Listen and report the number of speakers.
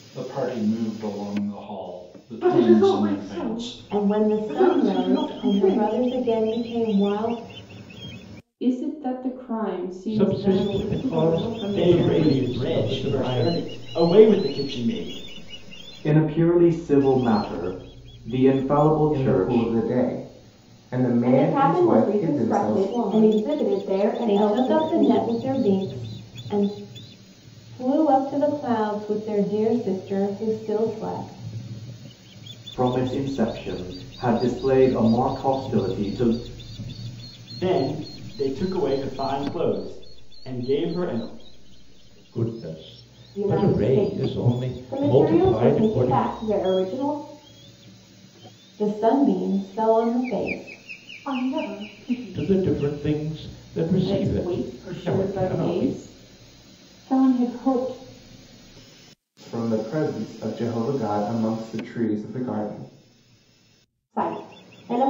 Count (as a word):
nine